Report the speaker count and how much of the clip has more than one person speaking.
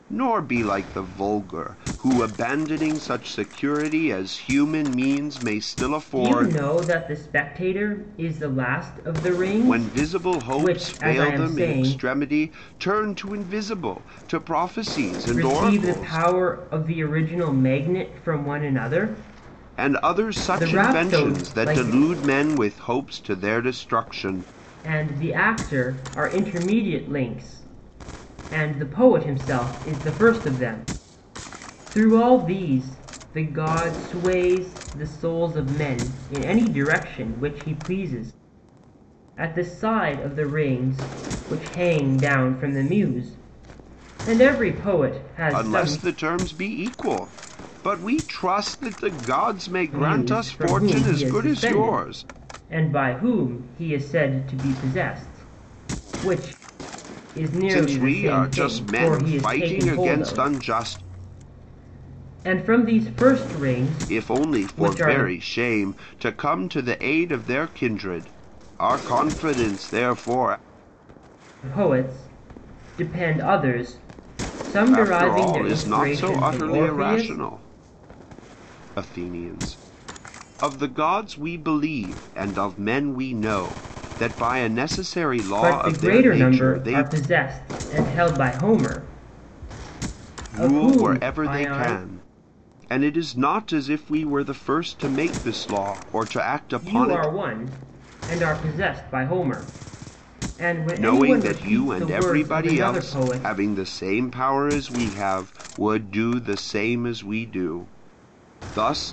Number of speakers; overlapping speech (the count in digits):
2, about 20%